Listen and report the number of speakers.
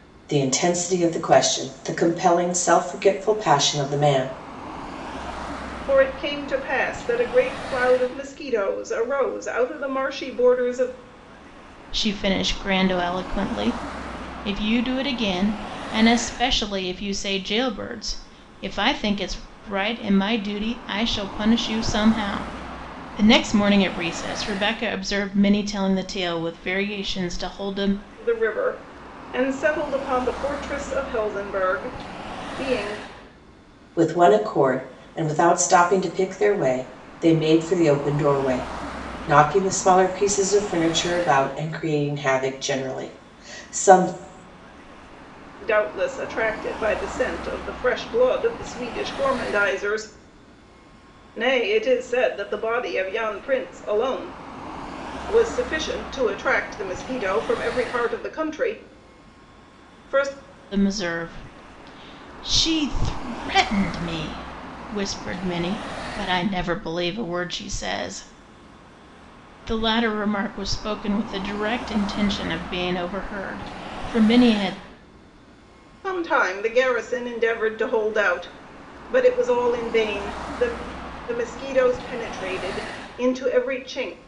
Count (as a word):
three